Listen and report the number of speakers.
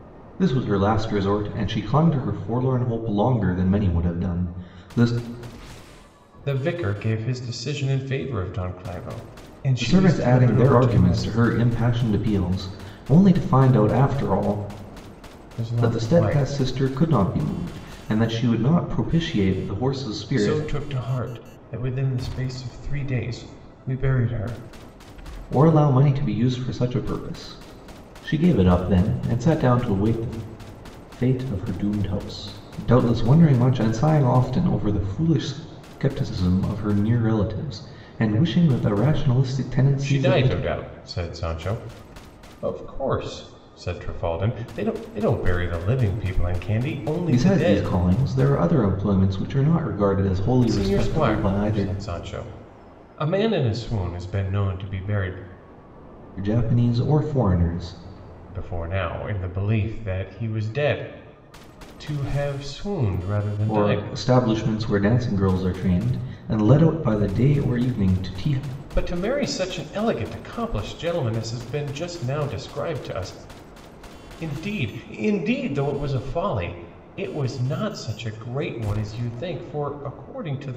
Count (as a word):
two